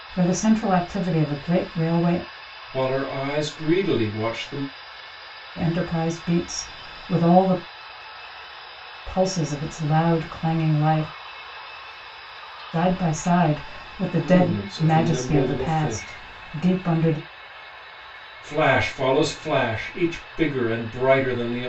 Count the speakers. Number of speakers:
2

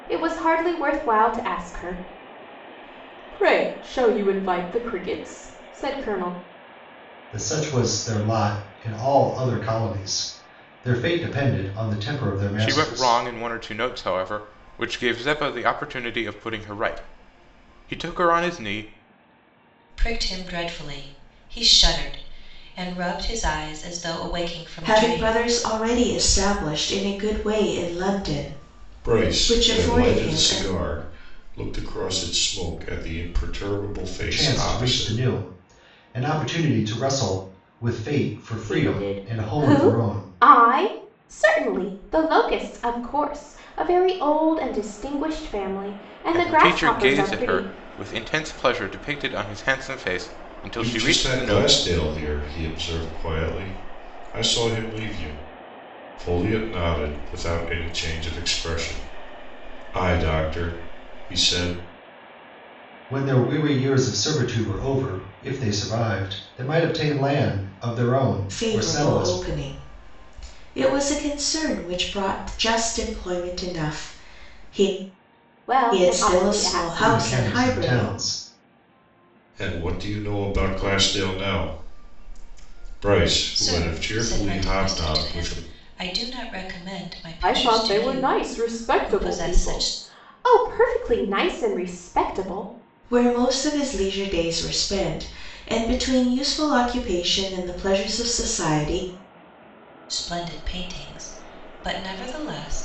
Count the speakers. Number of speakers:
6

